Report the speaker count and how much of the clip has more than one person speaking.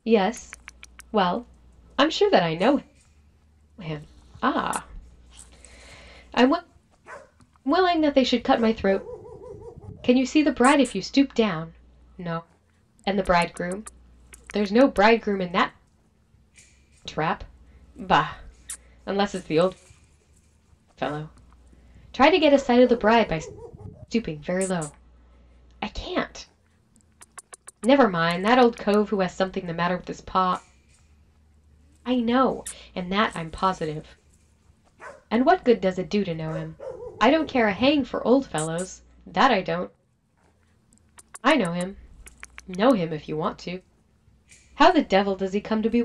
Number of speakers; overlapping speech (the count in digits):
1, no overlap